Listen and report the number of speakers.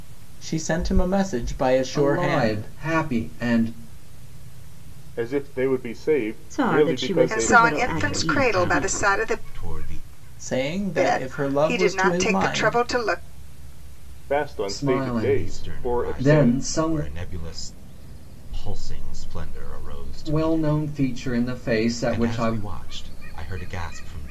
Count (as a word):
six